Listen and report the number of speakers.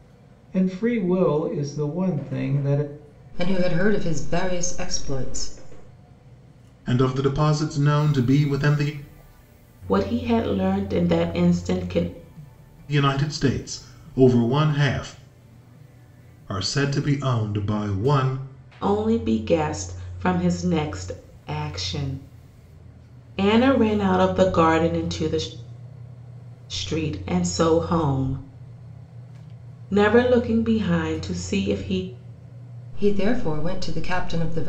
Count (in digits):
4